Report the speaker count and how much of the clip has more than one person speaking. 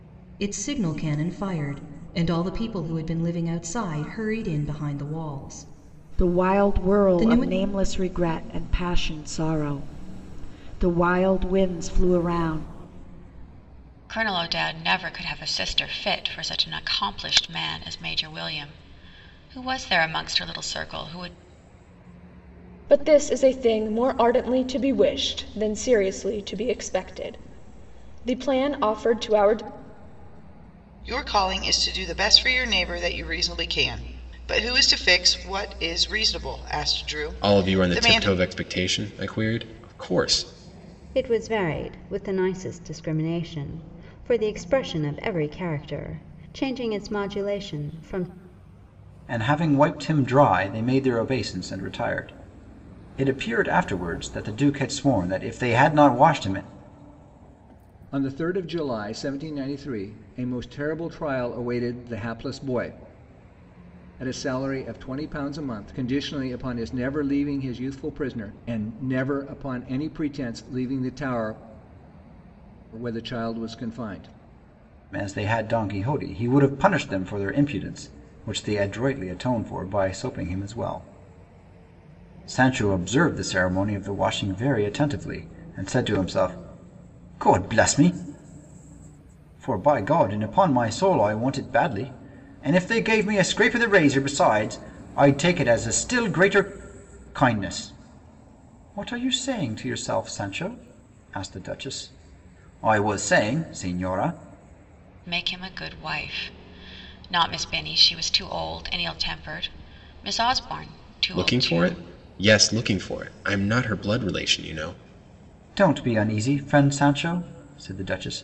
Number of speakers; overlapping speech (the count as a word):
nine, about 3%